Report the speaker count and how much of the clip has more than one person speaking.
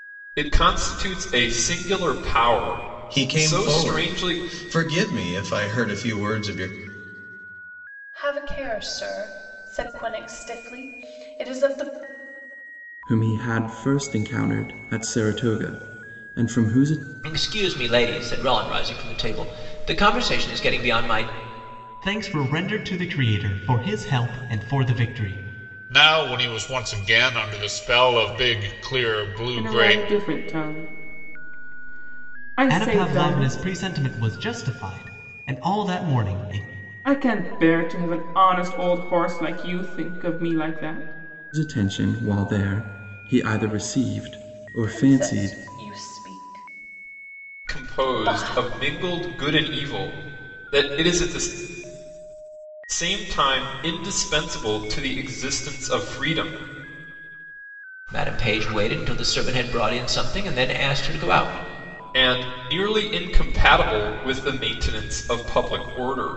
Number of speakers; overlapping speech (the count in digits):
8, about 7%